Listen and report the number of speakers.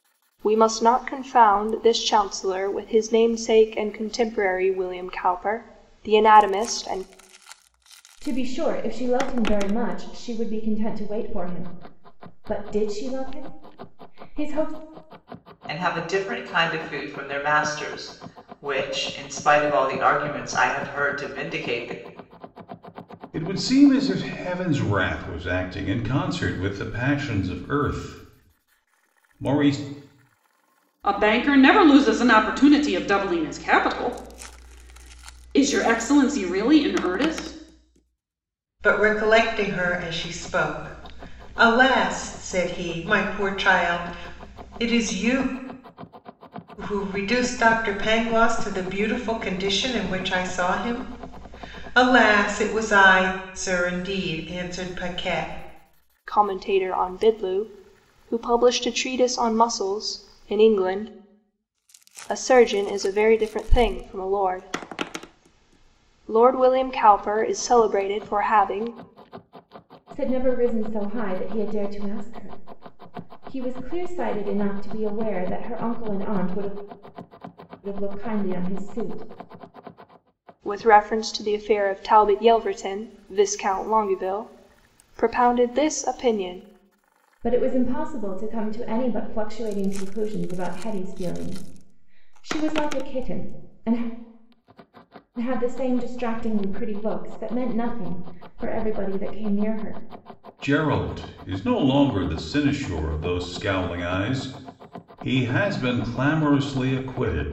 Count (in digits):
6